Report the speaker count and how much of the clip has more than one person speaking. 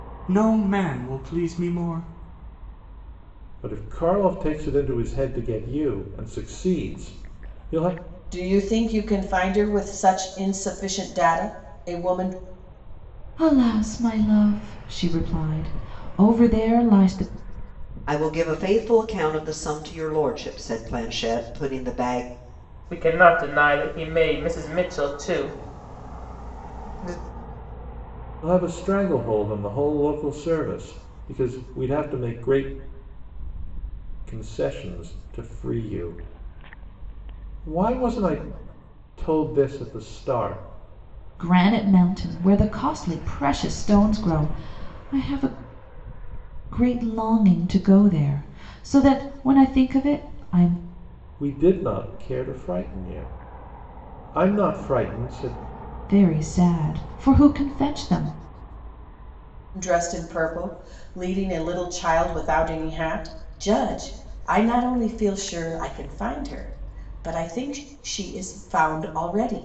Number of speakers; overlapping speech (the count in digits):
6, no overlap